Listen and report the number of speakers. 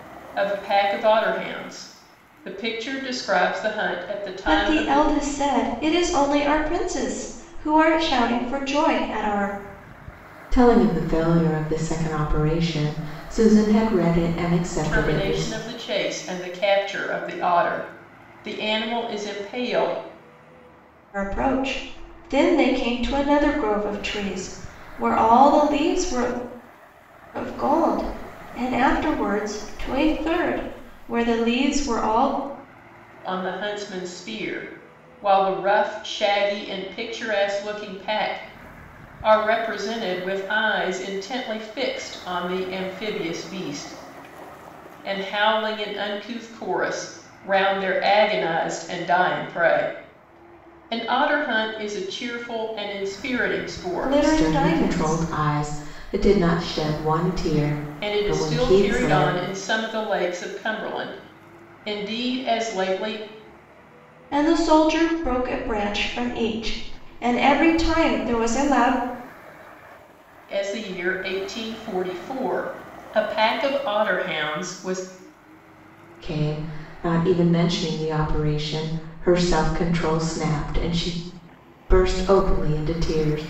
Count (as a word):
three